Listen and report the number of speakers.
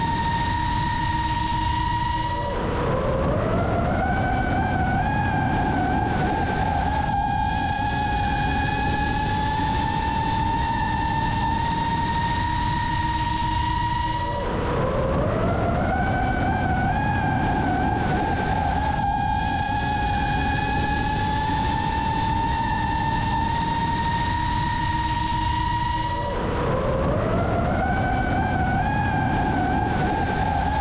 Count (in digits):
0